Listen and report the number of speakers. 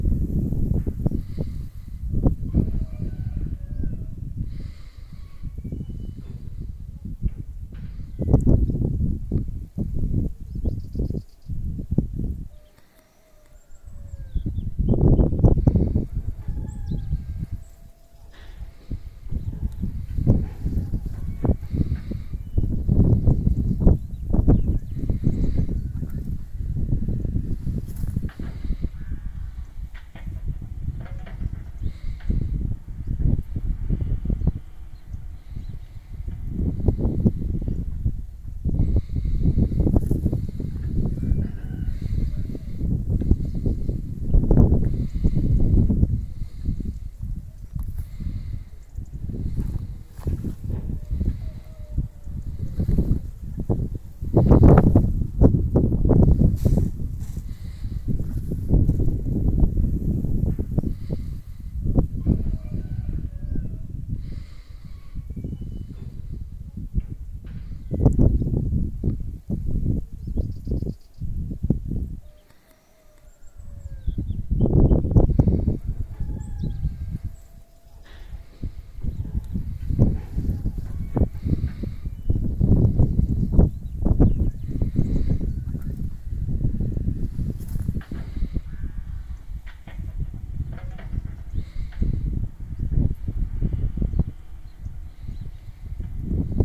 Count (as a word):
zero